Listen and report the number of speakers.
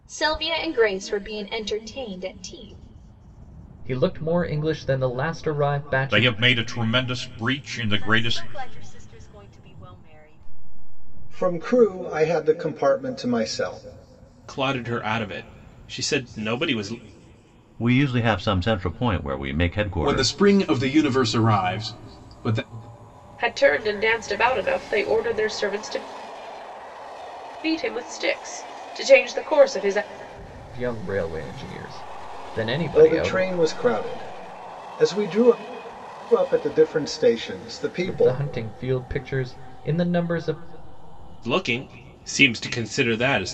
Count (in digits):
9